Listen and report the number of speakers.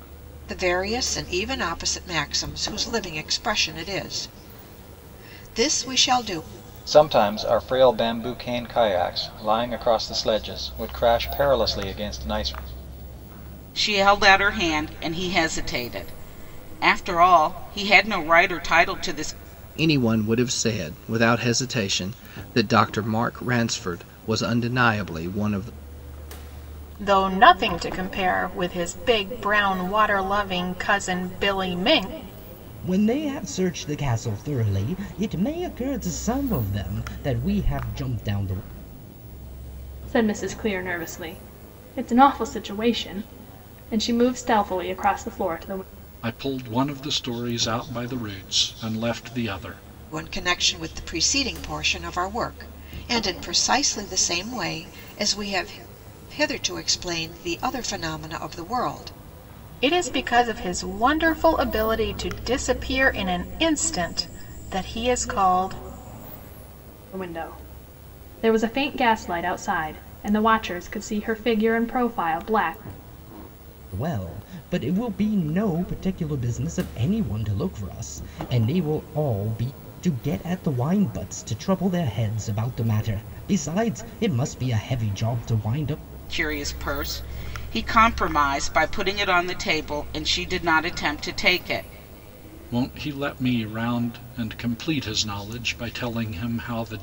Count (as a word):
eight